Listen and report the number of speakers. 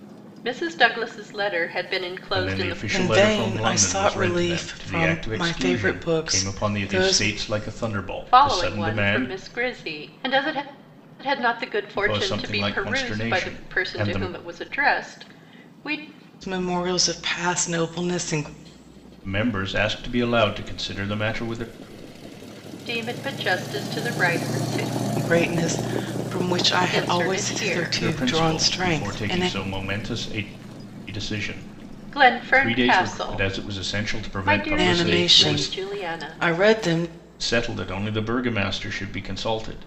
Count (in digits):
3